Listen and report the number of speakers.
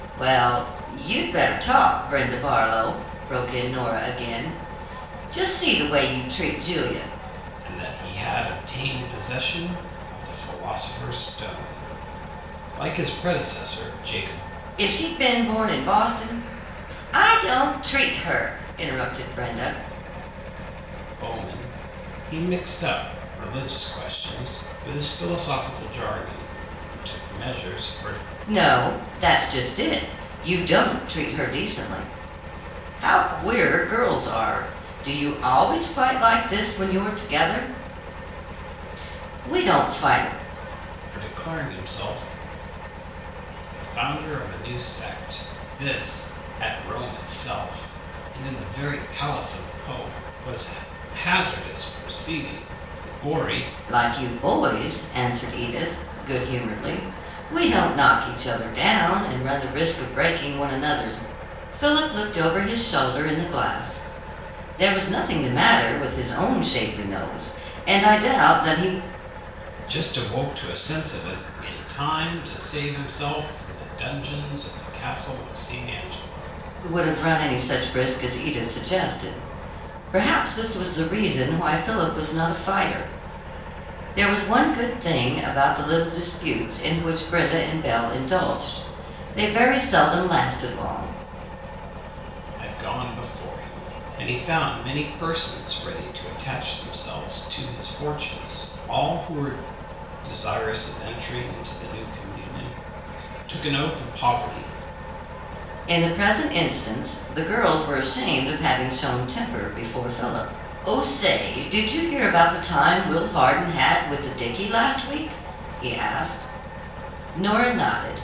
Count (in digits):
2